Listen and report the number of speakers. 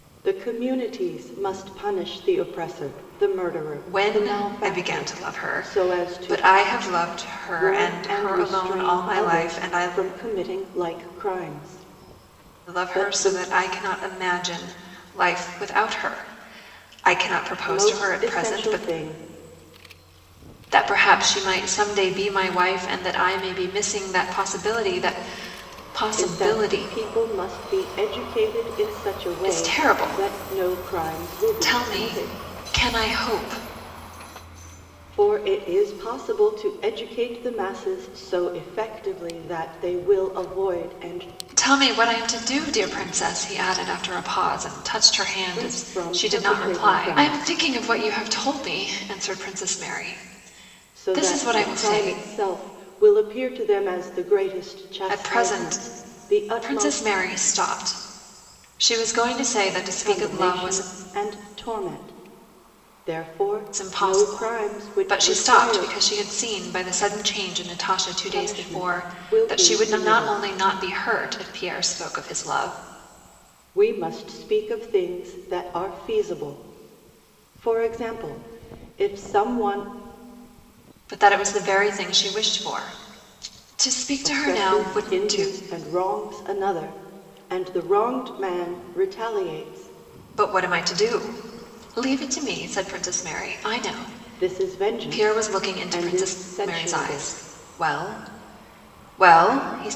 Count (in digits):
2